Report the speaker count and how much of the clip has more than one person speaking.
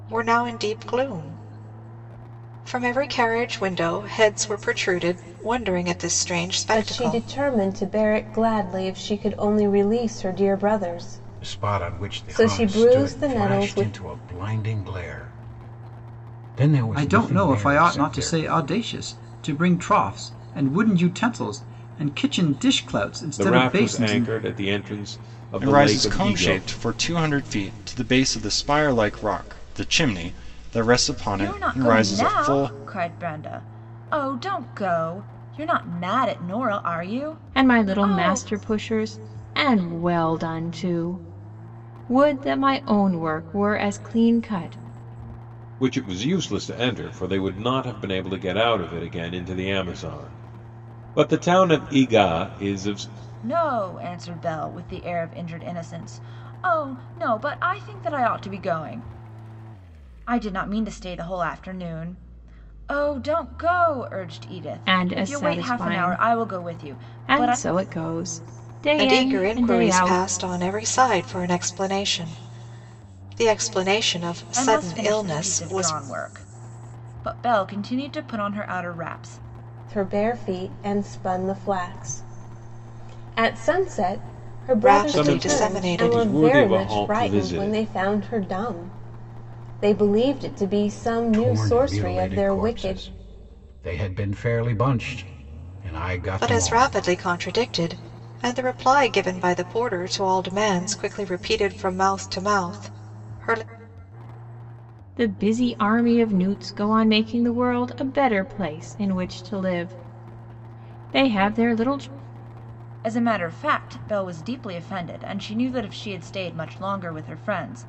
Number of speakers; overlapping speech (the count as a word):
eight, about 17%